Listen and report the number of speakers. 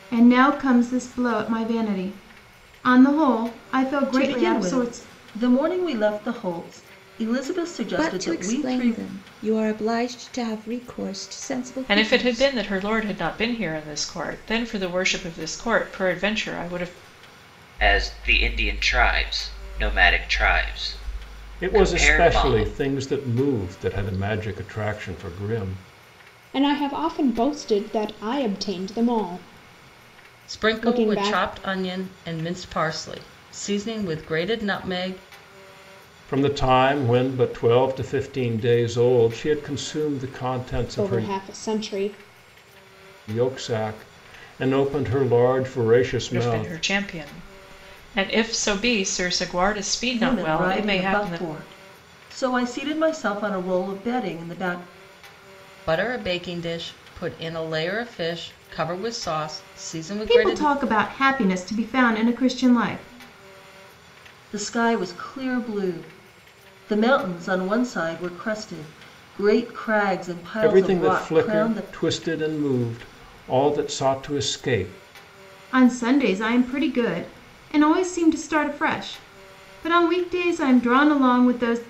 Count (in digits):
8